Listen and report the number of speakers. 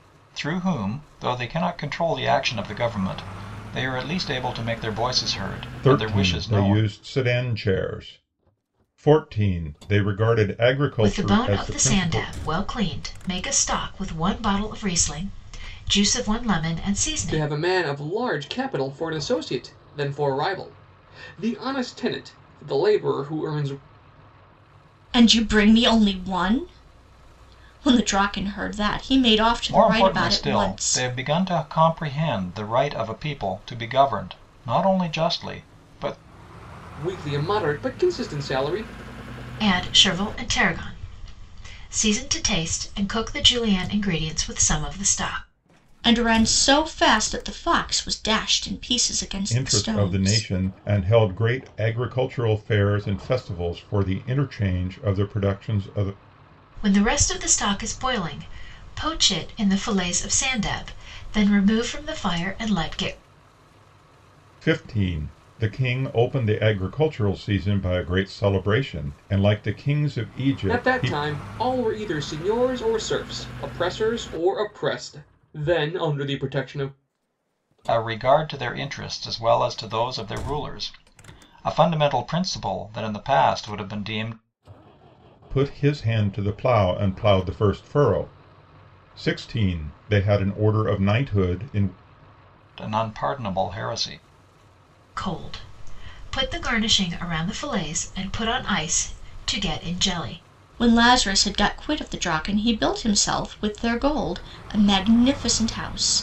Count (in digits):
5